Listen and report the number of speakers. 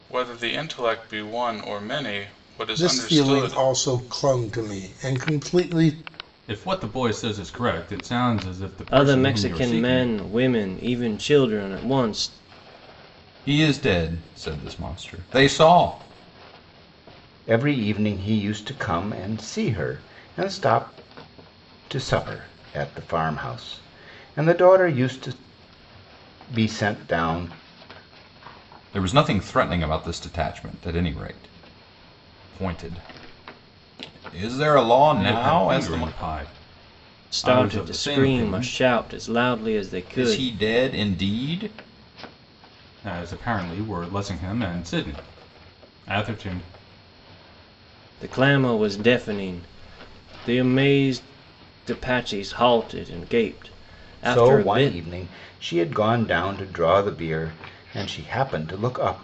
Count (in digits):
6